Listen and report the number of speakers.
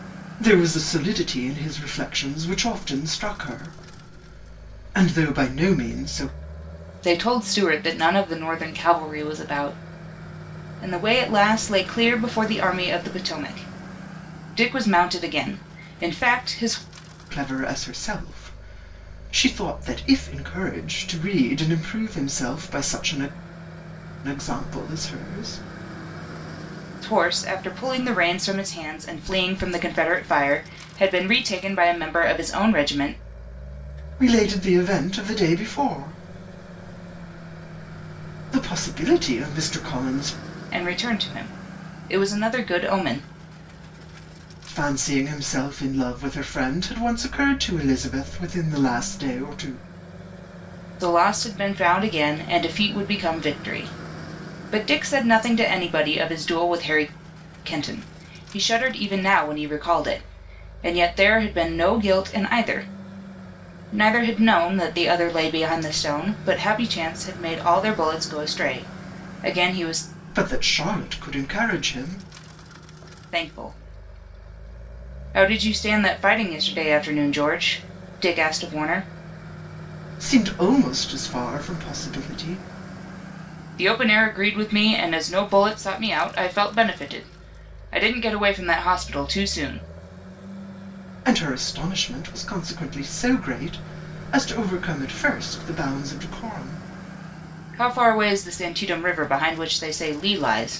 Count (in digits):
2